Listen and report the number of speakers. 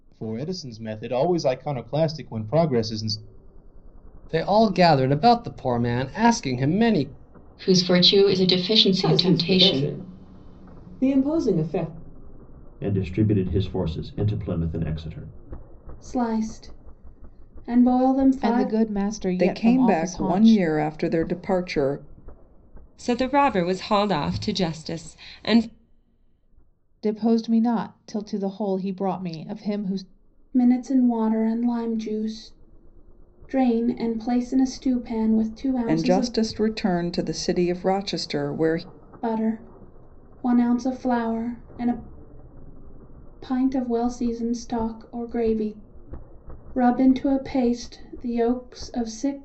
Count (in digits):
9